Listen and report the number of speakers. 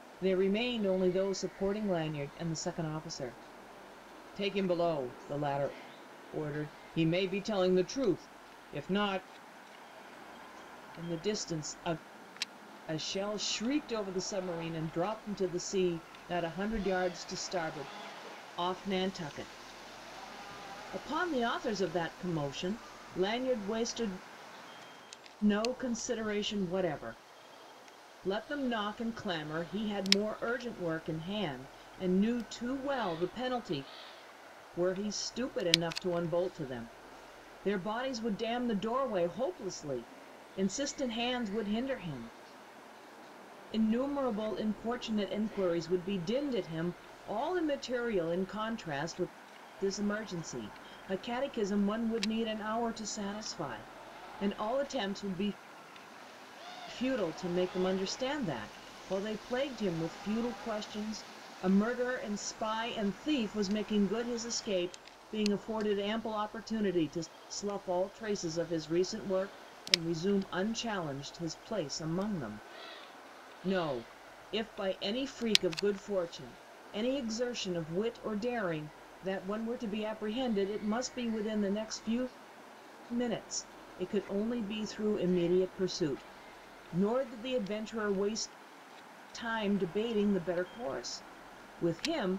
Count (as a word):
one